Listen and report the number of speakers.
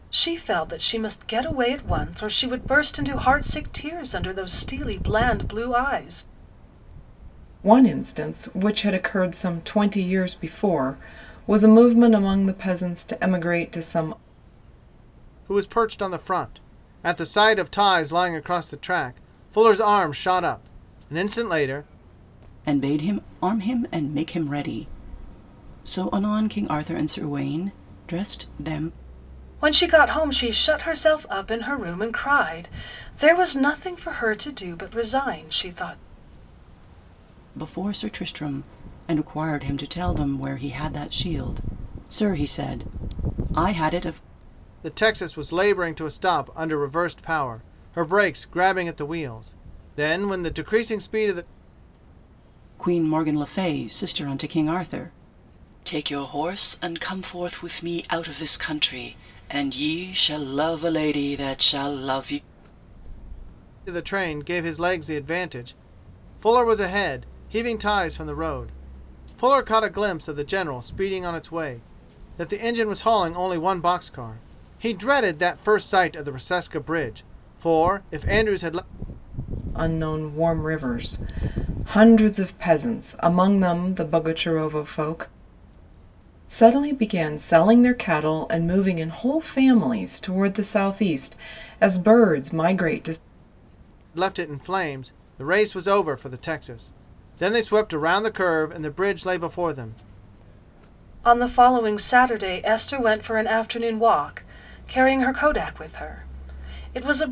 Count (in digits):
4